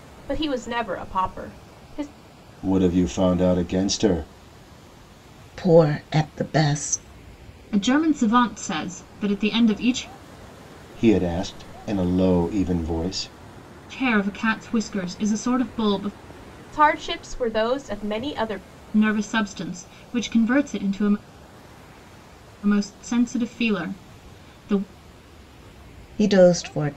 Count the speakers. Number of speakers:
4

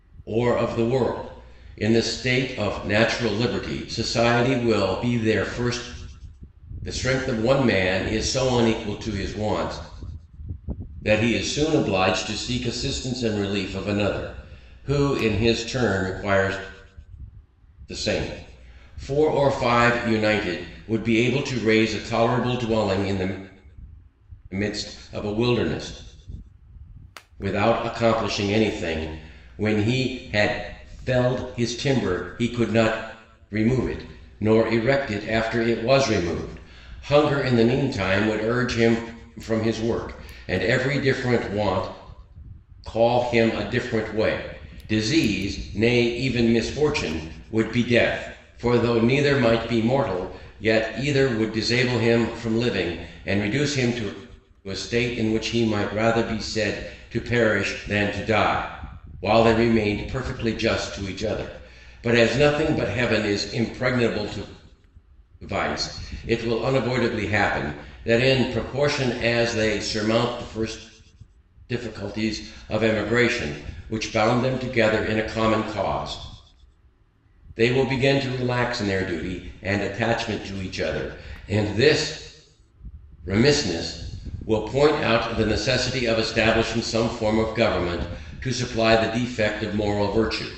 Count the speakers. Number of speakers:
1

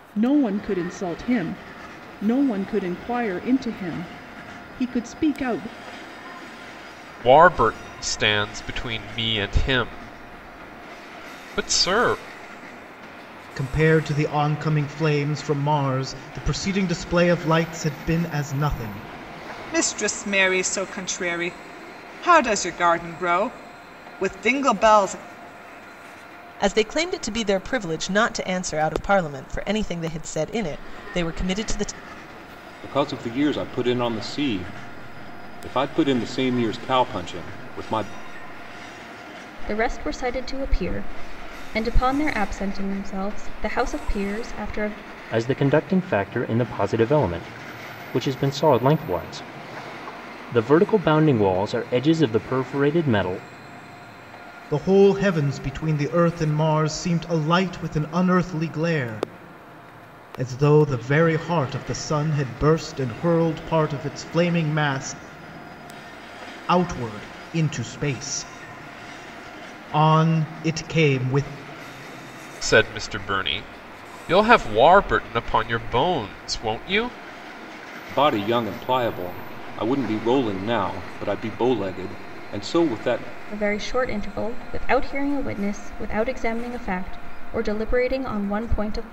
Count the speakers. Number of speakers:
8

